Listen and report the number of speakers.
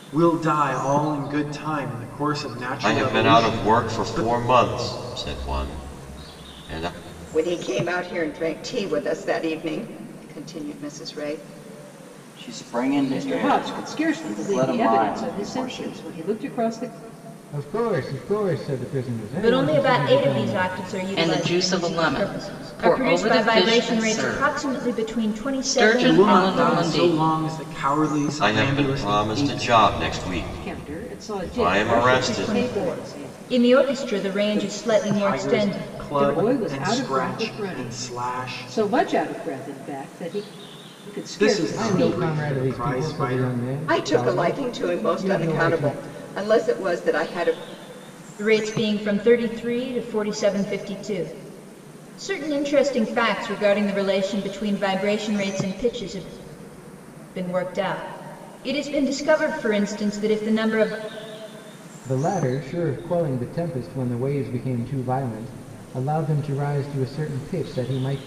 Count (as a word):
eight